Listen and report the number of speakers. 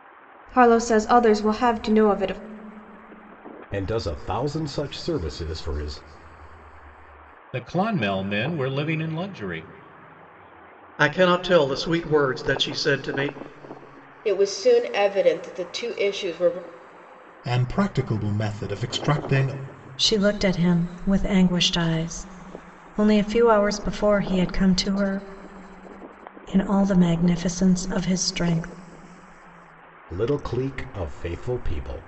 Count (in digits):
7